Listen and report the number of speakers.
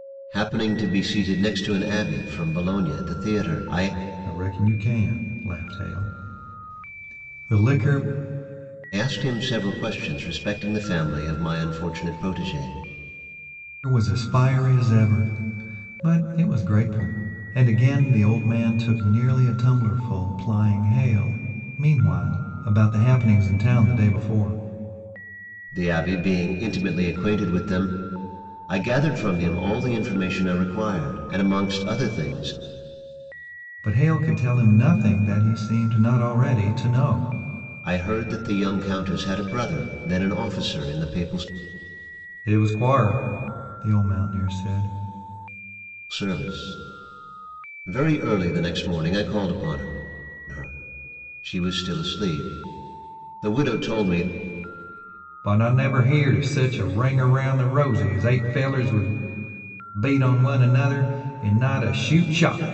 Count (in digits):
2